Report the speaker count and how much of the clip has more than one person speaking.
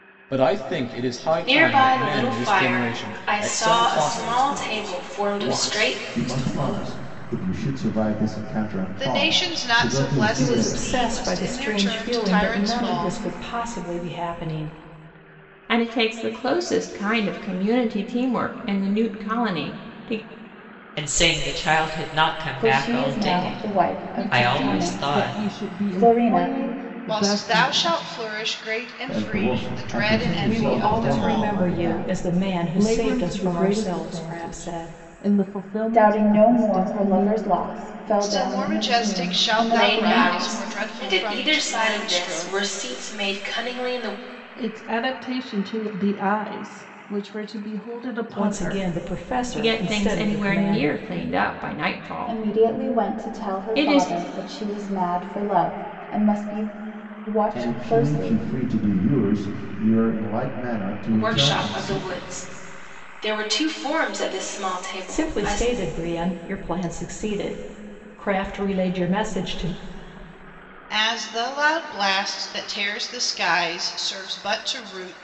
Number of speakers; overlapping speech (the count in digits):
10, about 43%